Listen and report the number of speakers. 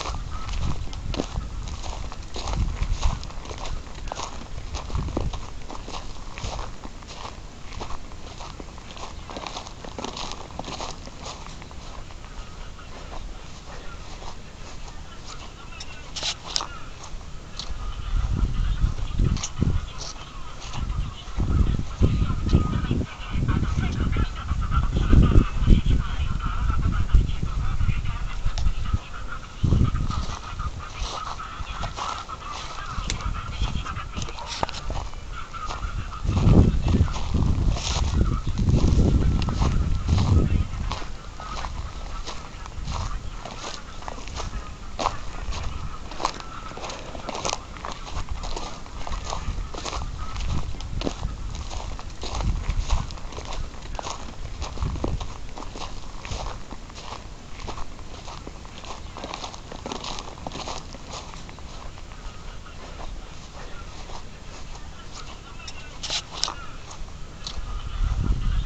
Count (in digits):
0